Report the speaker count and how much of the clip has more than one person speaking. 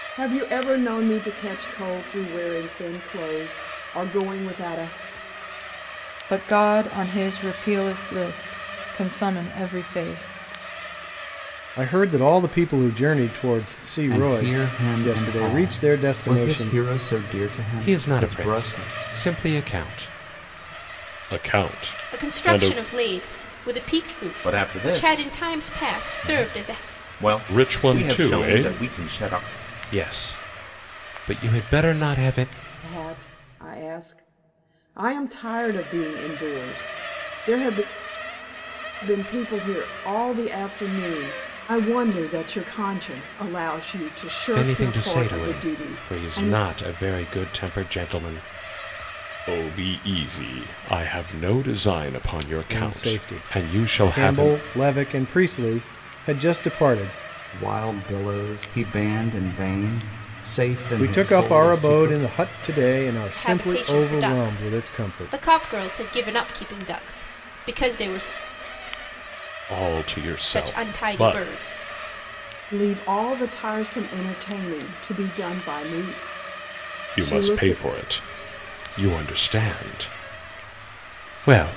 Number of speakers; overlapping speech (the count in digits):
7, about 22%